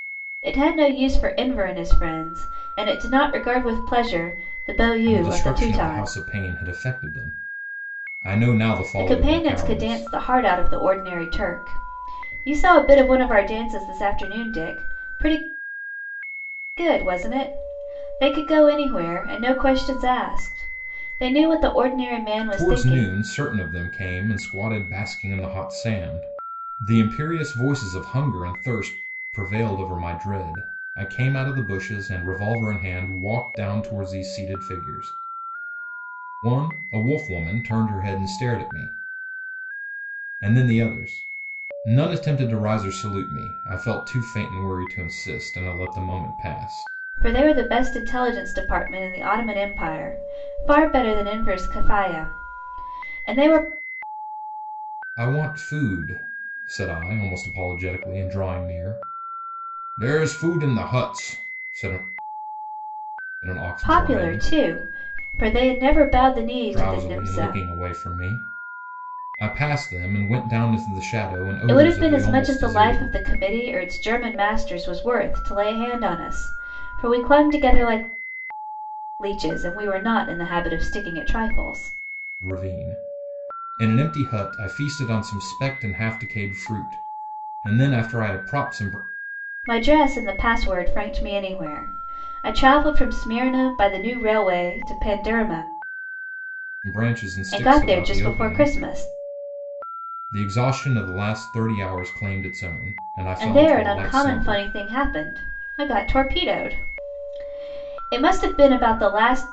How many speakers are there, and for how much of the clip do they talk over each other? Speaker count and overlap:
two, about 8%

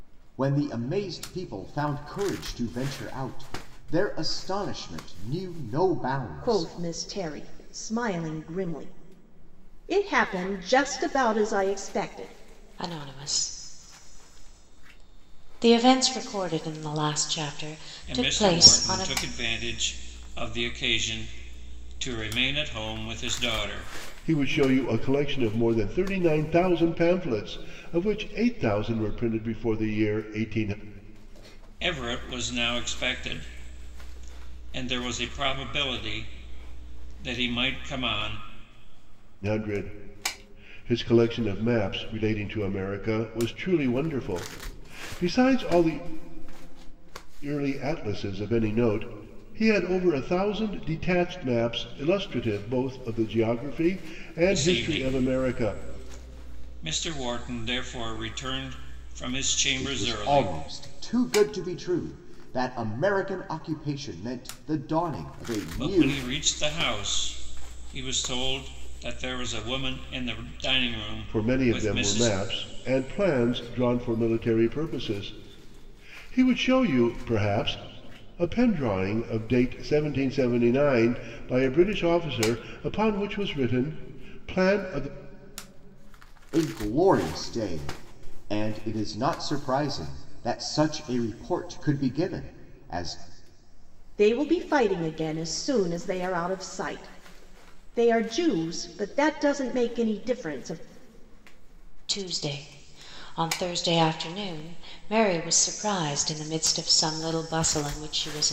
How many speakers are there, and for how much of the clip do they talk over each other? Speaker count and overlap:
five, about 5%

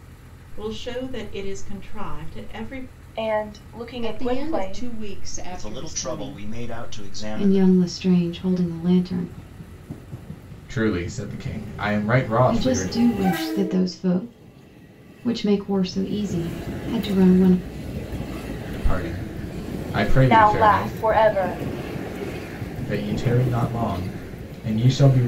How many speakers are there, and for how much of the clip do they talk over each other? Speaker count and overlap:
six, about 14%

